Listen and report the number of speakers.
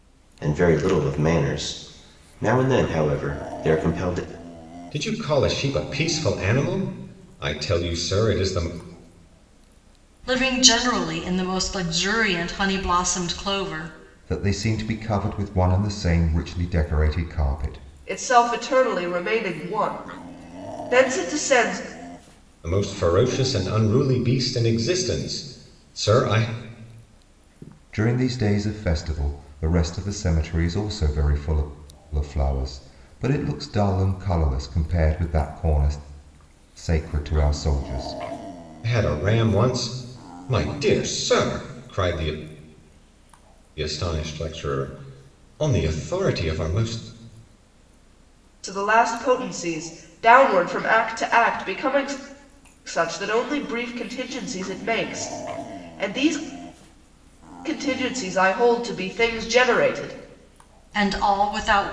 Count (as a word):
five